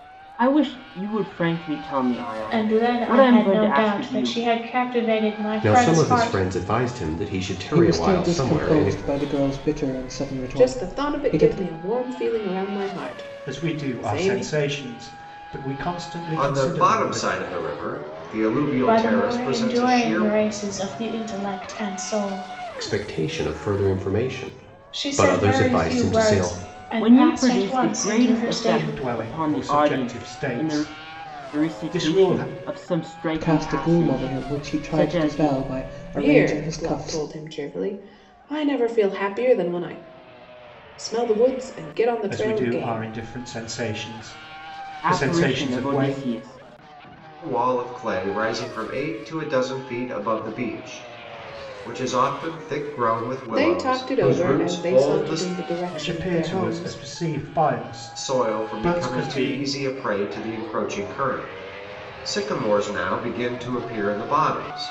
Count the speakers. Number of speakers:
seven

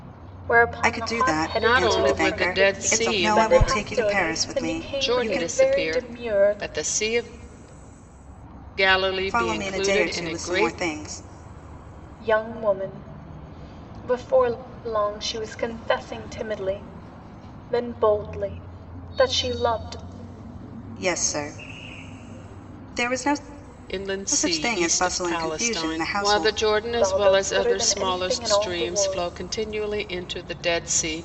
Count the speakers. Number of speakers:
three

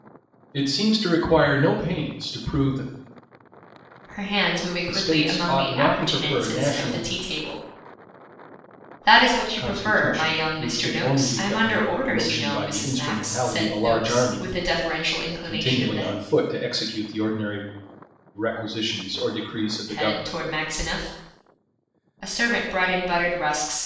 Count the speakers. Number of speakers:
two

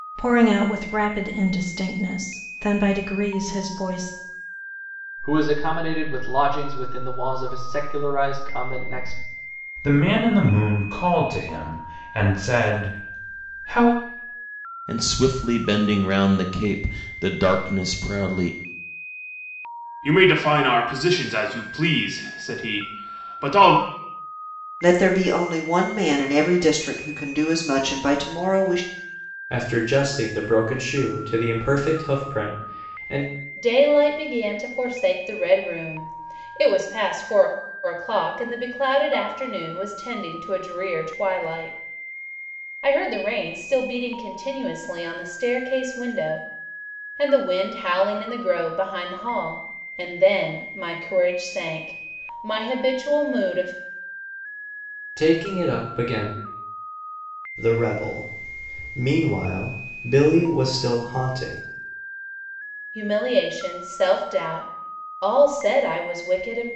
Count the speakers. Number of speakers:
eight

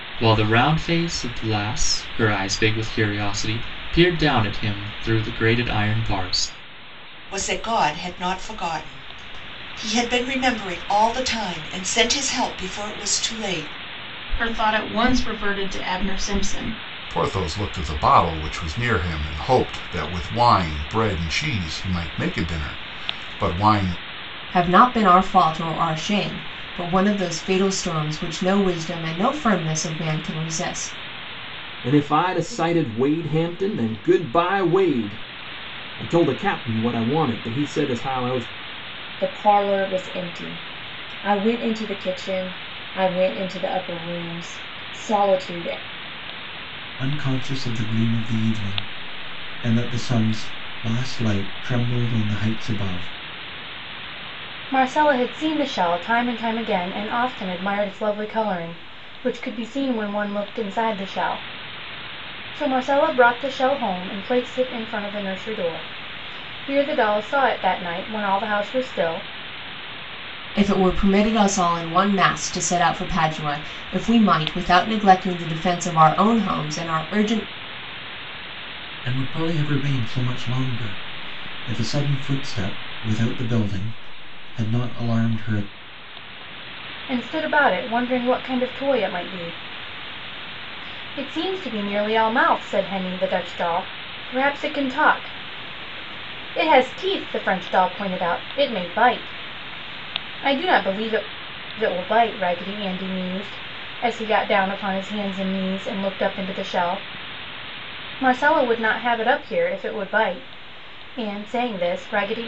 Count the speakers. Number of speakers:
nine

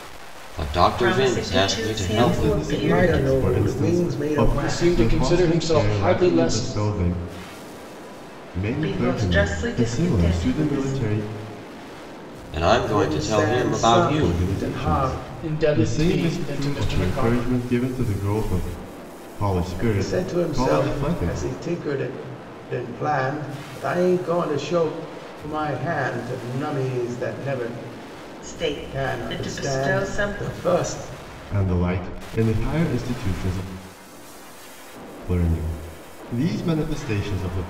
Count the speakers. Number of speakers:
five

